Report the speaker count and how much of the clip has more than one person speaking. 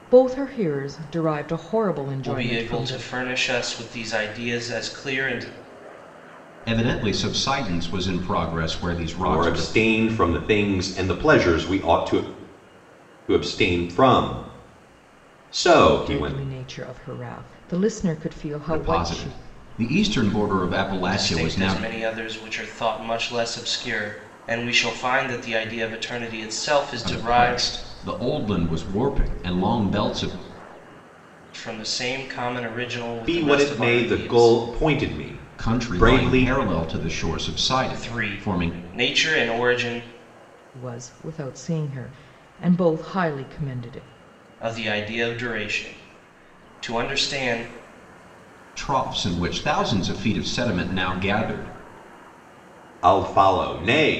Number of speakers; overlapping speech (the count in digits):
4, about 13%